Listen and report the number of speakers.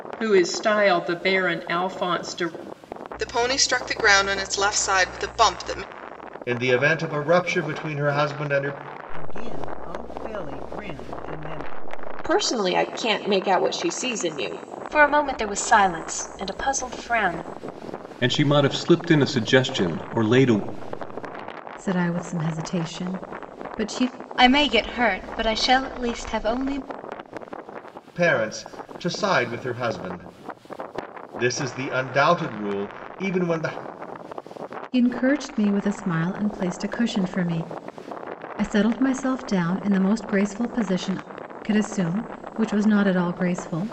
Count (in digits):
9